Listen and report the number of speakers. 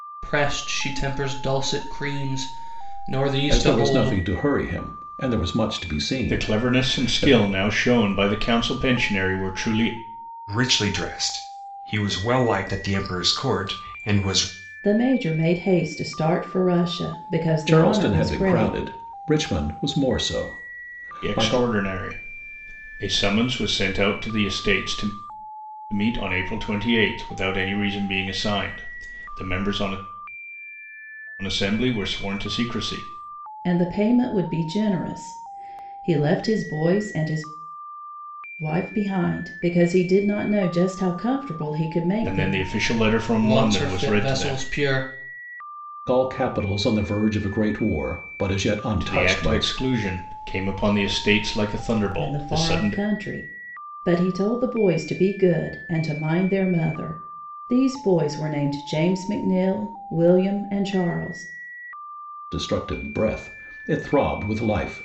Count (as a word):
five